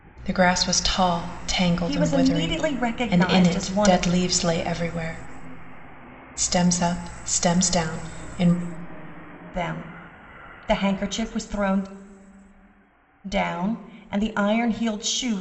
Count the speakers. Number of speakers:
2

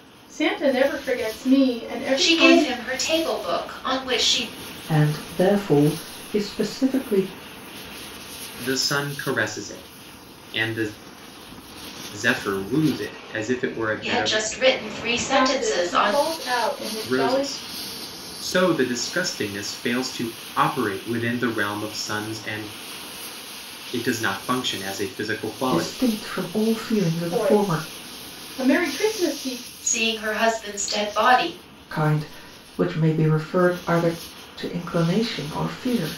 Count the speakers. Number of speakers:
4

